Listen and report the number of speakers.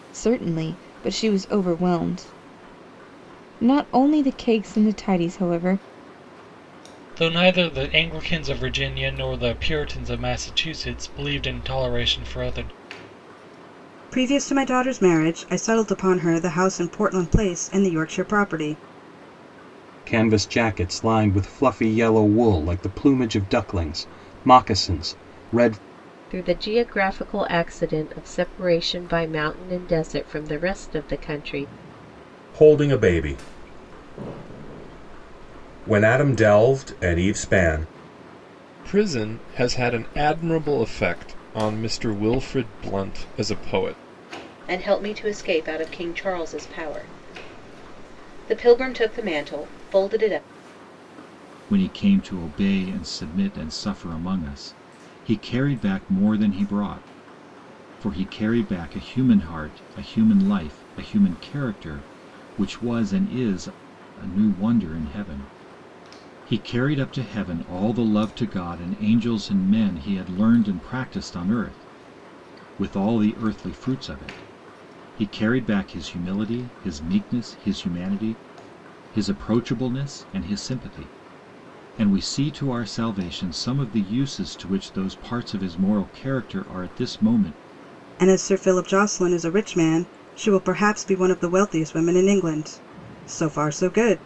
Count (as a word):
nine